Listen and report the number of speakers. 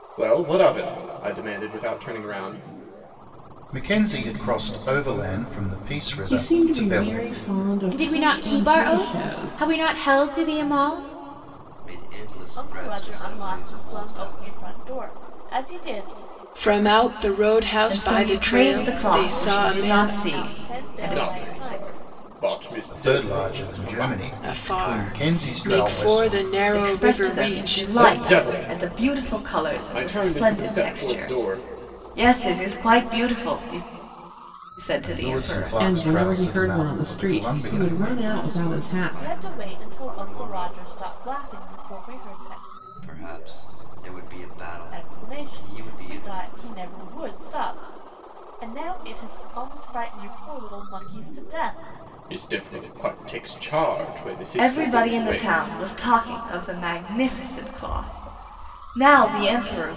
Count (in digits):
8